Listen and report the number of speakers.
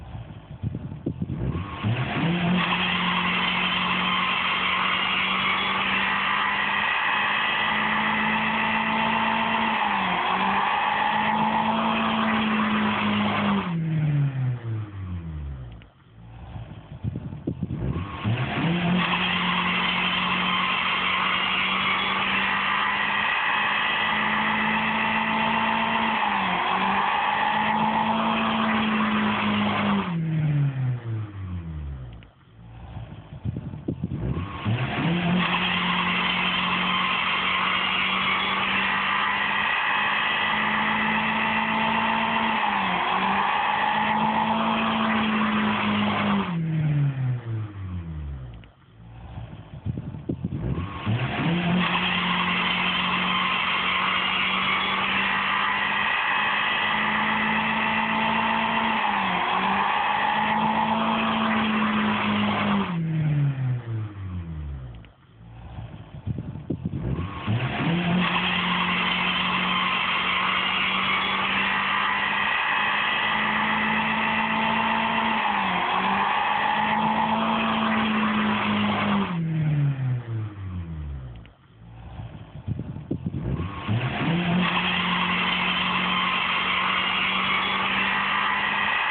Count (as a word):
zero